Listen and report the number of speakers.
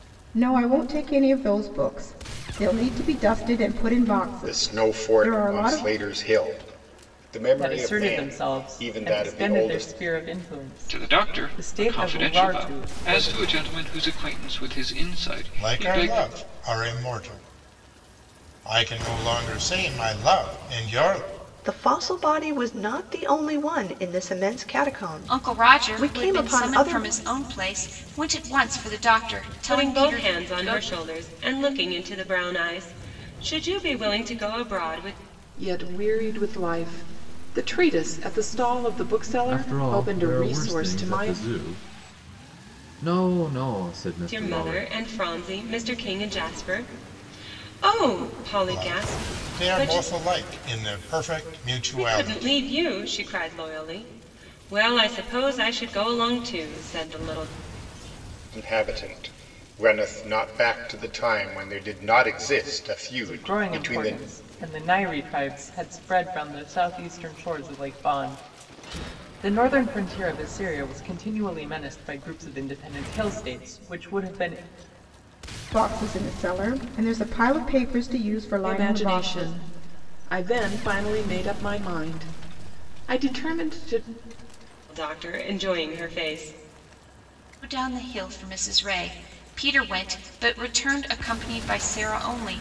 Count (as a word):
ten